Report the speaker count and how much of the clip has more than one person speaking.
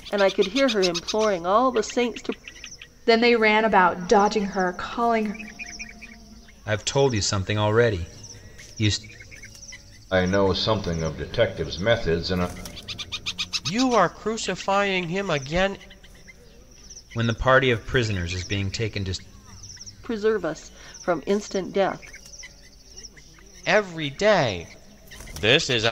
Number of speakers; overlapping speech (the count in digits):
5, no overlap